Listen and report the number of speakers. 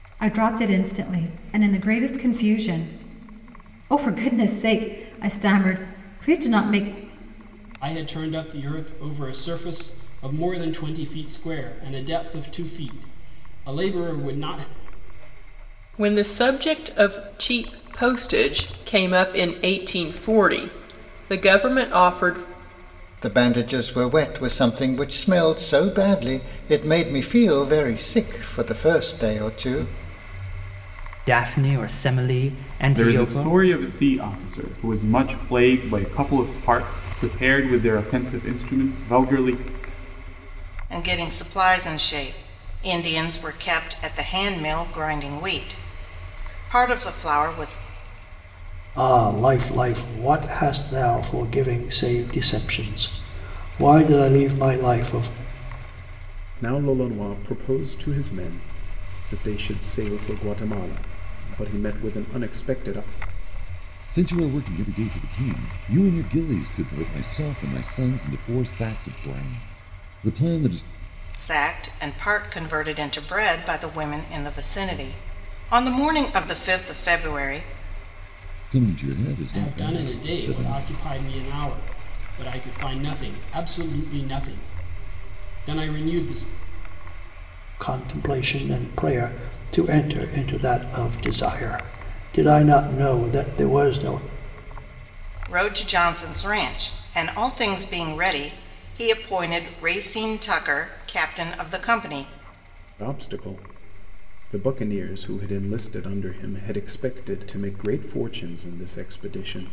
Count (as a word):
ten